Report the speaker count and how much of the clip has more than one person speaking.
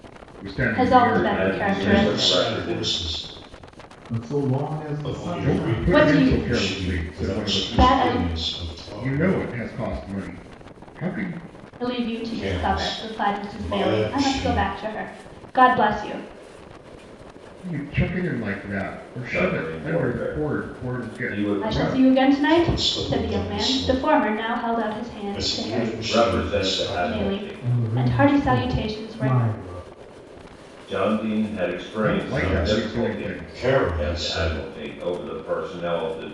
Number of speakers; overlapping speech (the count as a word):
five, about 53%